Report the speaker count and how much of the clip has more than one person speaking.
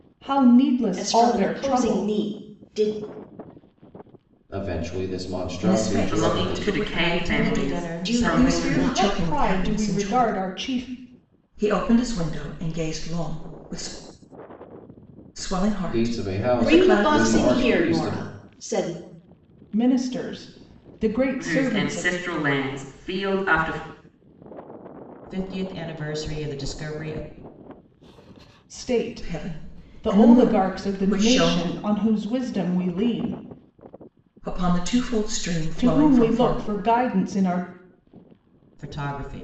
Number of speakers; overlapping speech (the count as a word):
six, about 32%